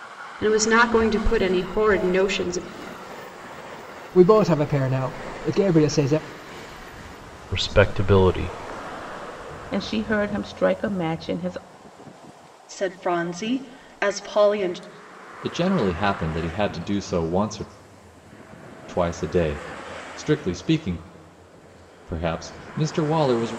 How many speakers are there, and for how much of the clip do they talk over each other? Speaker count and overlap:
6, no overlap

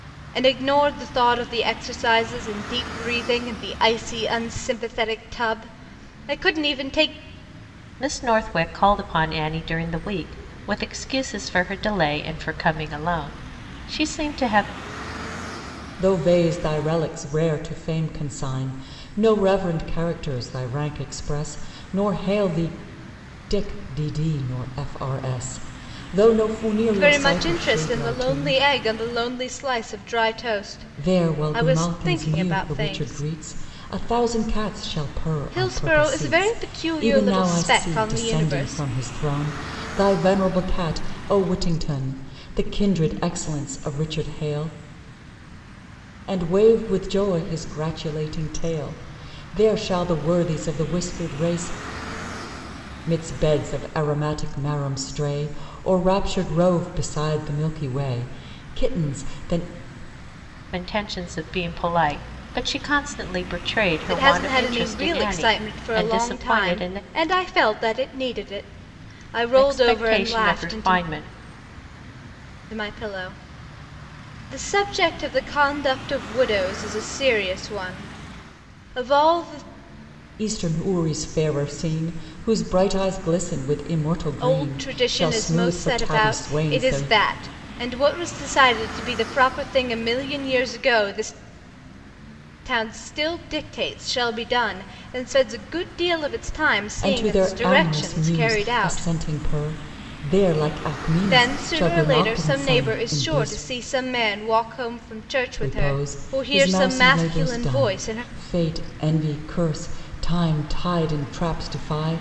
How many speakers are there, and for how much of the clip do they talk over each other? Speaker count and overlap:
3, about 19%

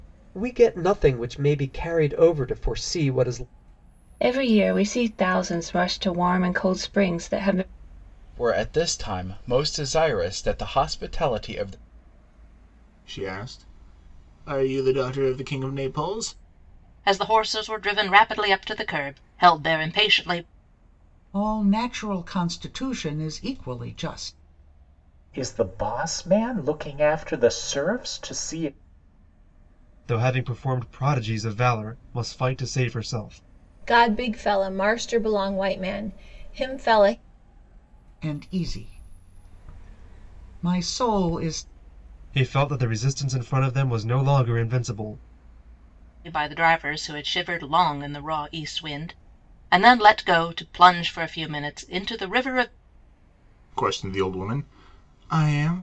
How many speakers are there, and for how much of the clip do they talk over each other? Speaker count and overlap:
9, no overlap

